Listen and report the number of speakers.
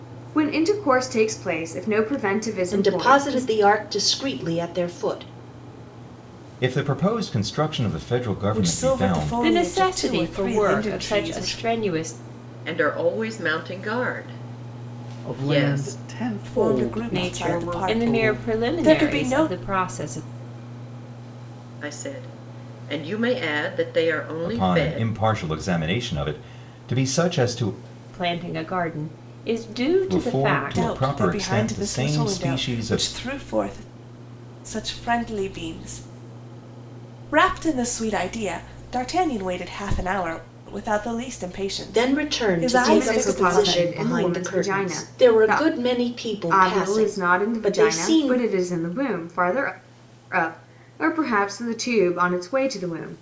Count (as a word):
seven